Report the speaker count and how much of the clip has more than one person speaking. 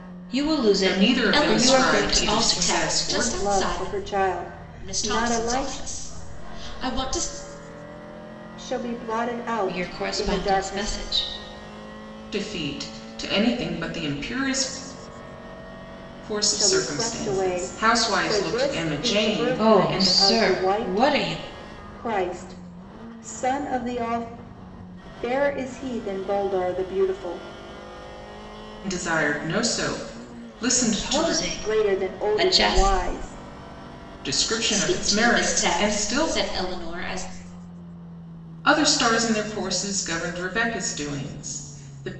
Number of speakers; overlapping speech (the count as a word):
four, about 33%